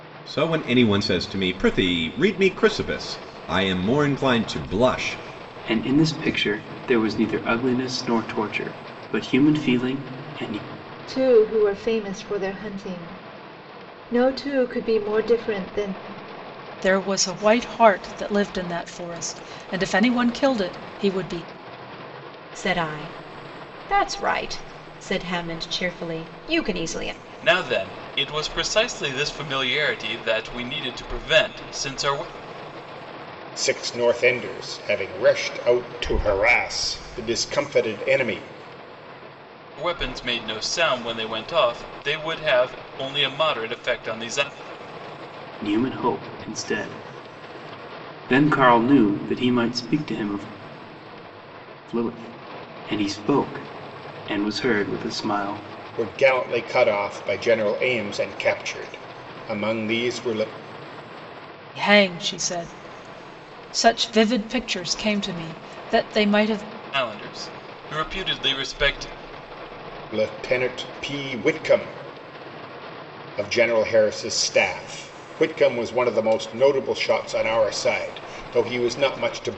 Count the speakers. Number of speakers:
seven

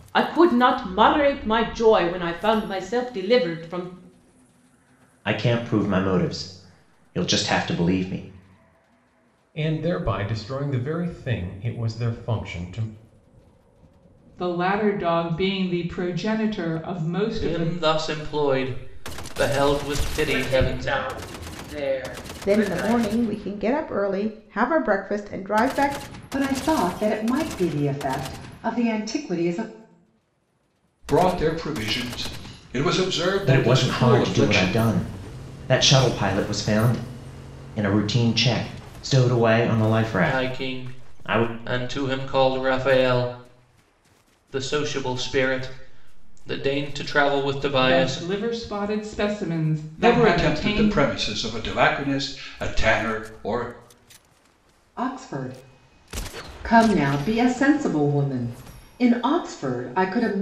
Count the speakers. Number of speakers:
nine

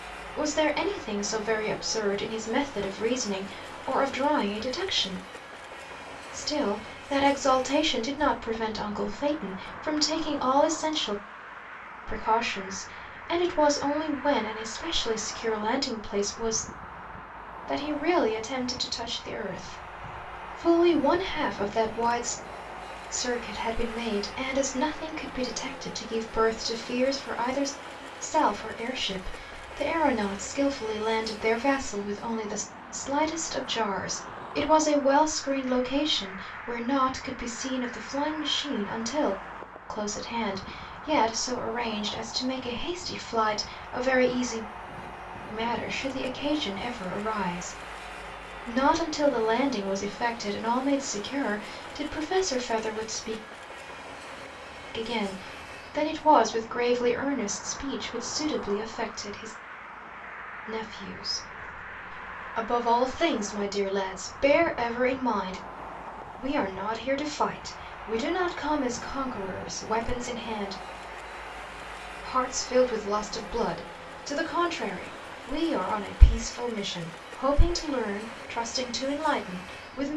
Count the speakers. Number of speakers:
one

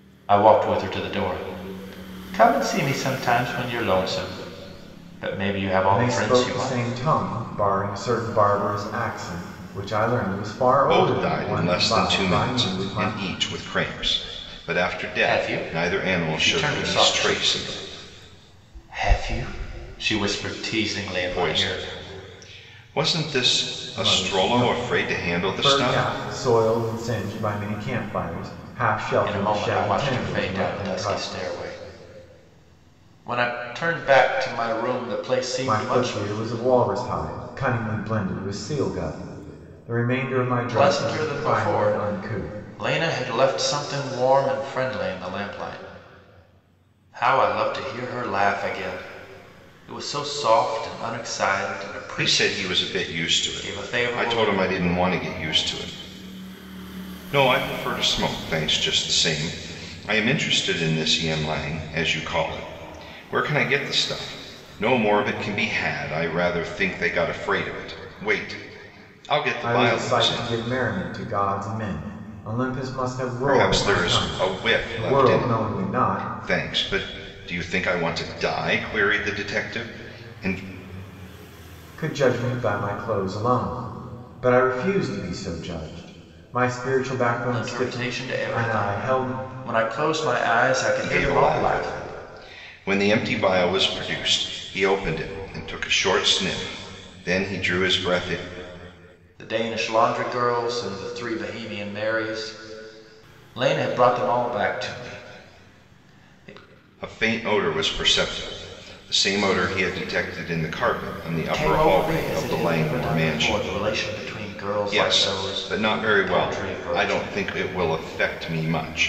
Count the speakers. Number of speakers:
three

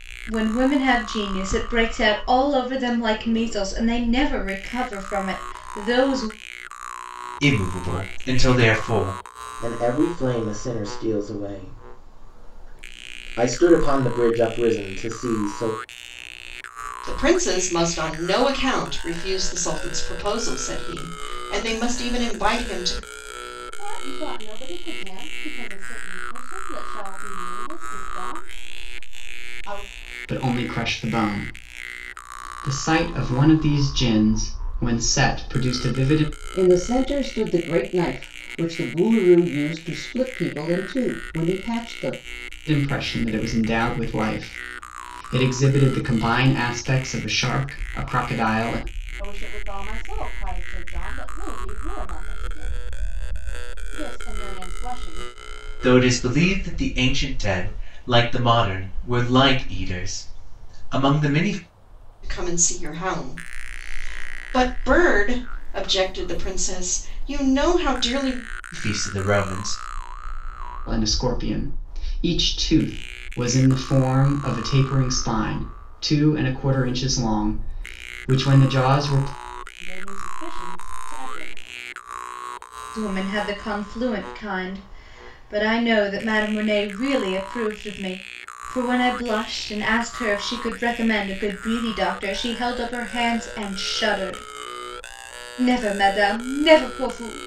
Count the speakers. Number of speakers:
seven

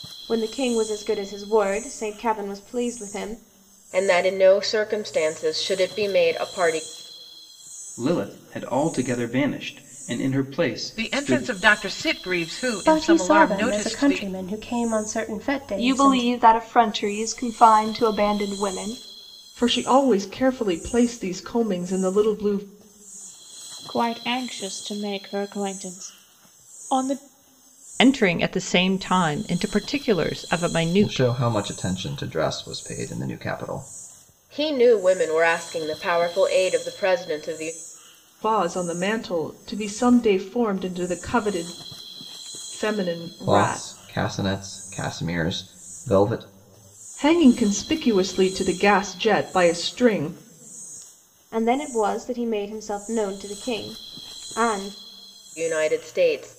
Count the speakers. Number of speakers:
ten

